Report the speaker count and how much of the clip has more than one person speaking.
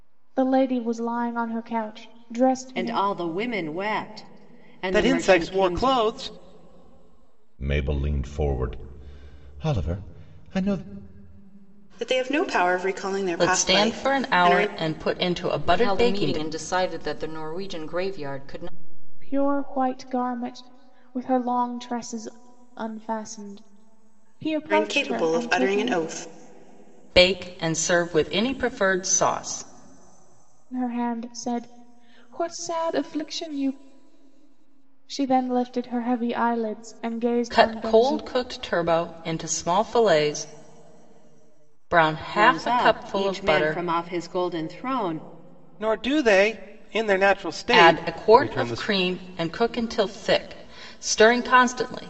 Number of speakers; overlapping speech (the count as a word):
seven, about 16%